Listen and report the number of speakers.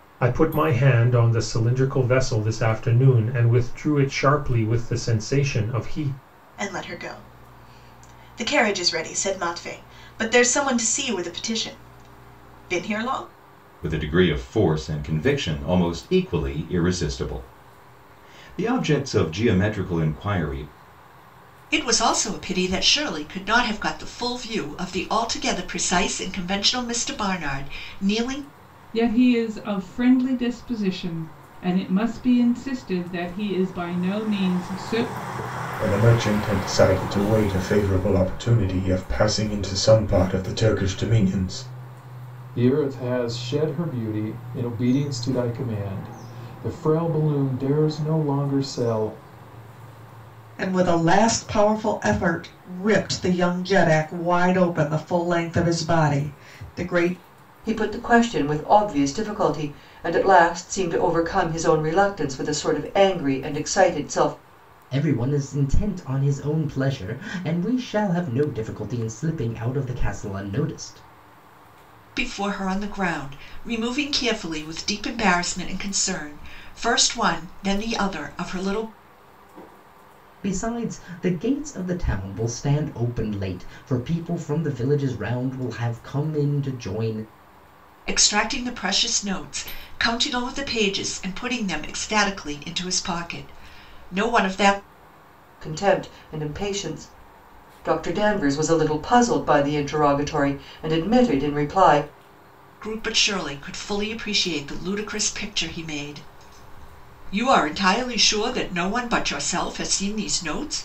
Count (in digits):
10